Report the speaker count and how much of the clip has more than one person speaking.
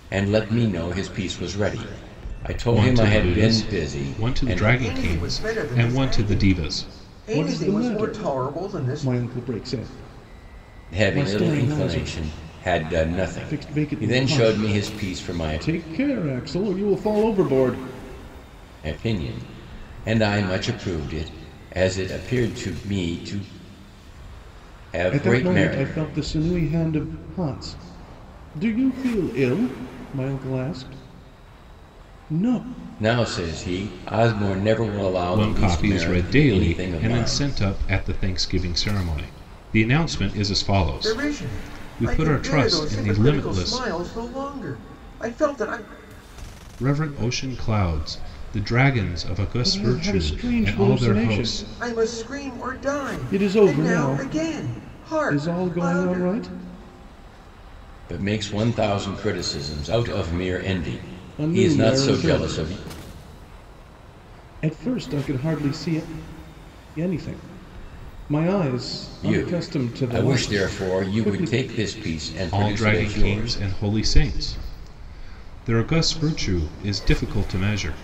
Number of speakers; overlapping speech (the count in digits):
4, about 33%